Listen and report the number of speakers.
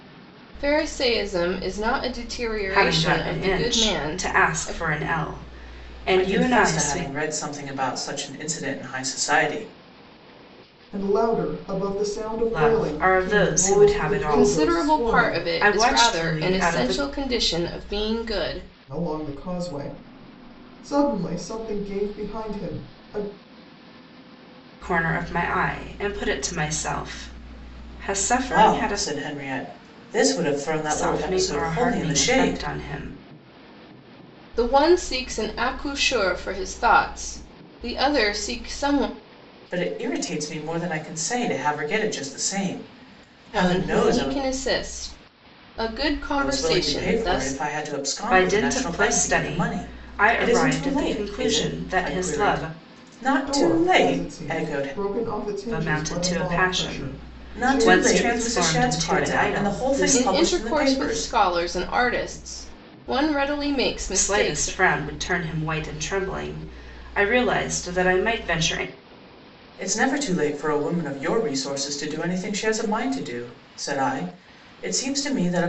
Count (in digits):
4